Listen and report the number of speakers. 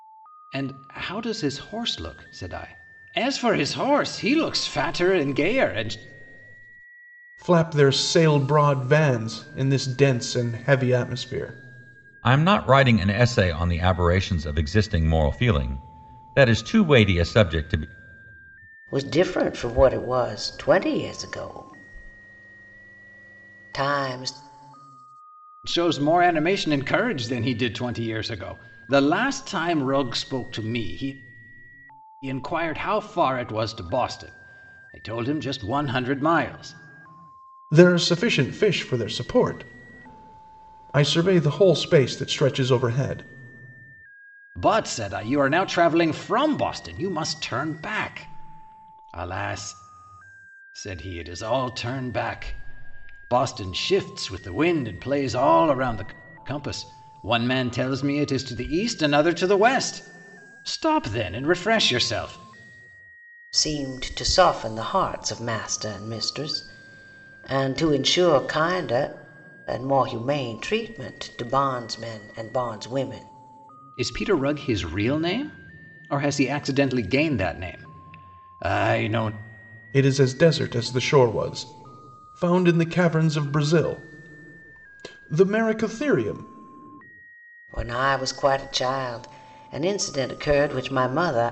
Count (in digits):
4